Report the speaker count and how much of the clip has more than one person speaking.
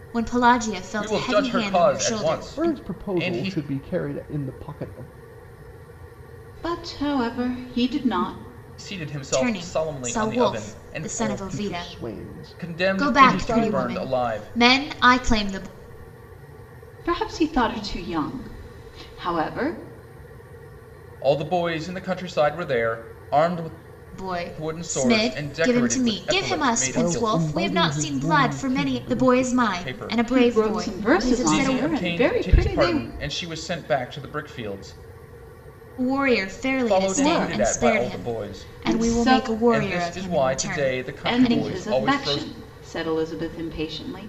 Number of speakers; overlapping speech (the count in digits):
4, about 47%